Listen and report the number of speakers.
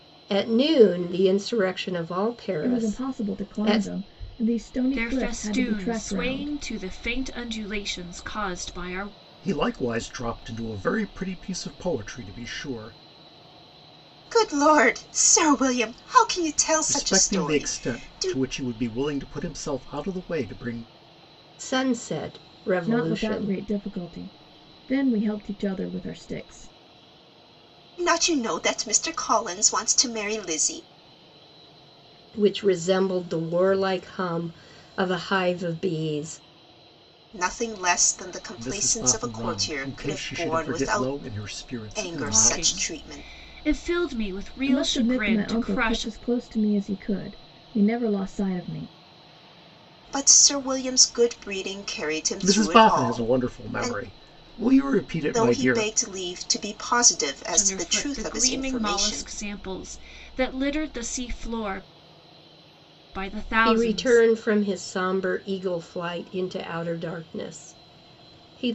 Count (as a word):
five